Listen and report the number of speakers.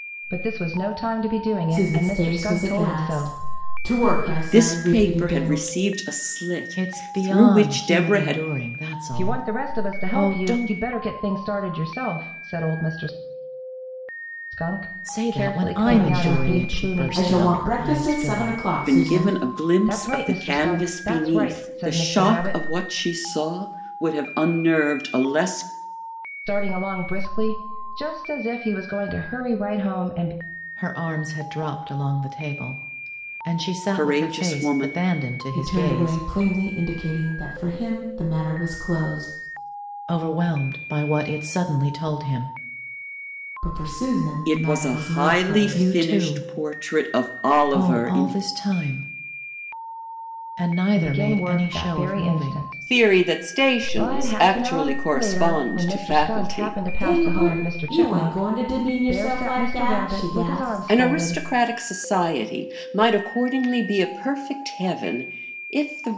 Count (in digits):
4